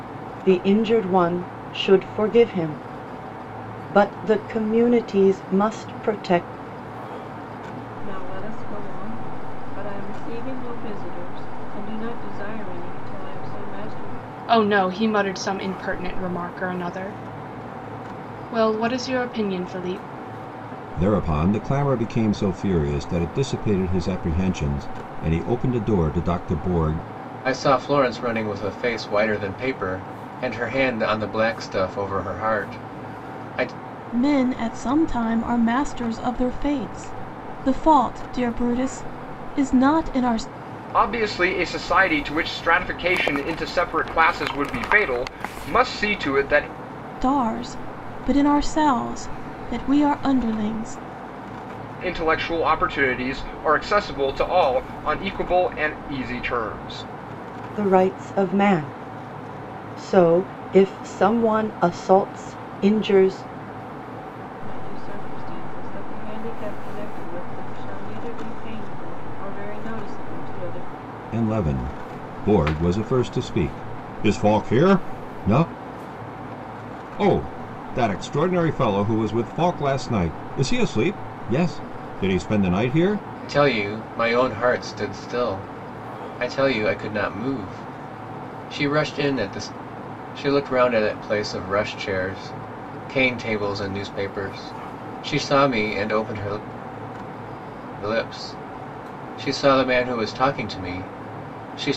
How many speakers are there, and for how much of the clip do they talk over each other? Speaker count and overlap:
seven, no overlap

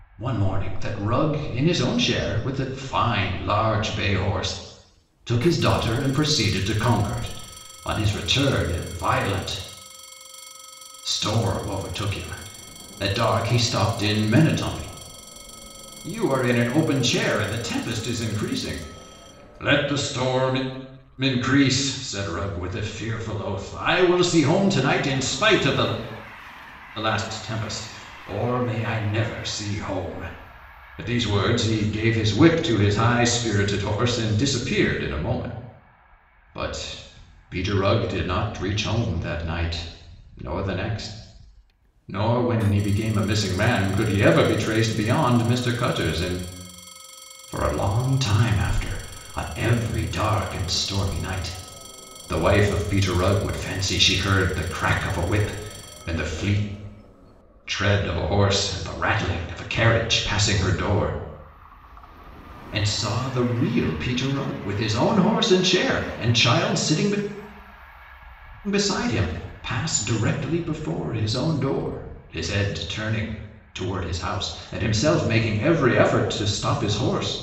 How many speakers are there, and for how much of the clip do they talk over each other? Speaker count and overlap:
one, no overlap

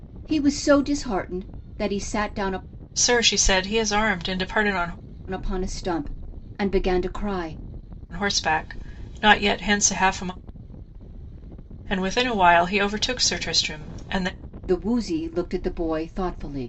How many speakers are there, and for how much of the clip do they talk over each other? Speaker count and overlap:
two, no overlap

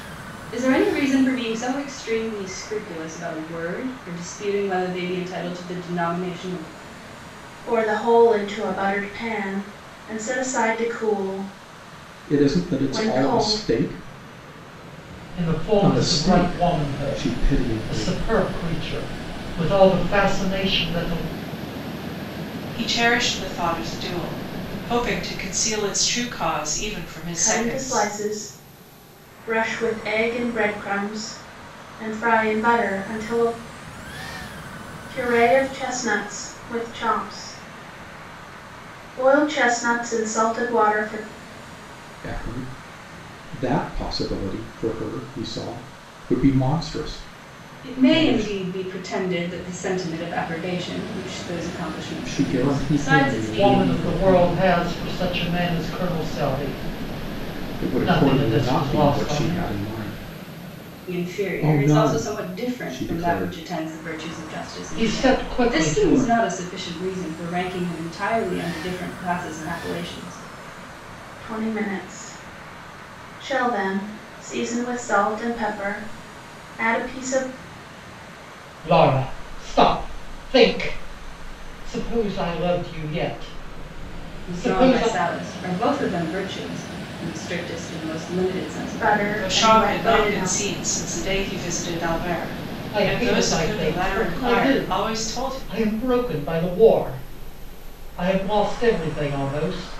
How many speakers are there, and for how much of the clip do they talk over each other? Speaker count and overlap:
five, about 19%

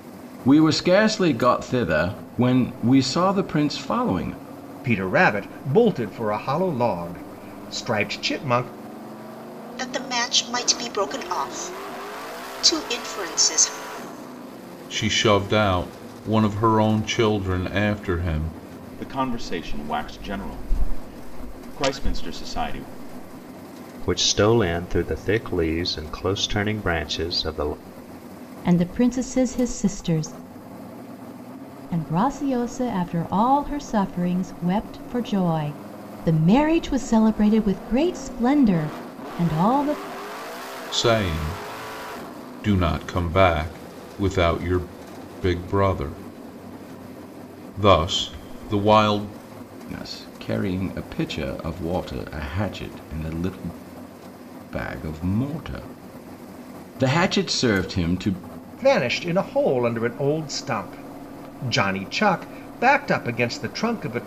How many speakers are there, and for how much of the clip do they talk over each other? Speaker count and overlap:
seven, no overlap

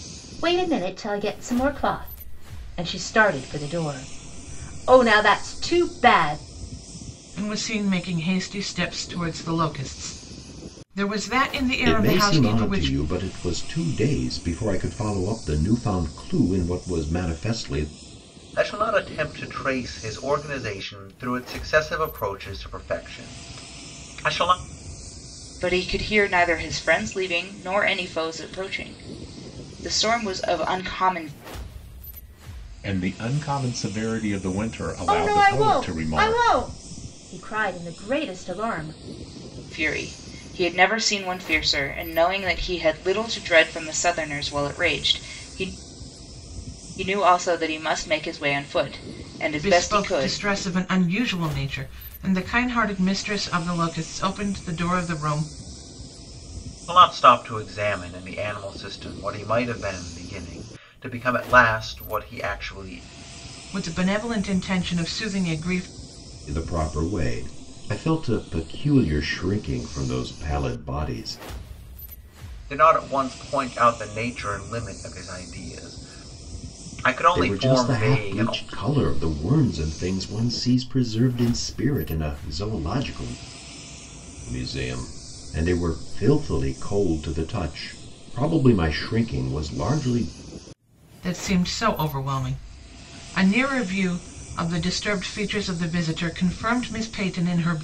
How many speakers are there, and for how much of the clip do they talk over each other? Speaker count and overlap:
six, about 5%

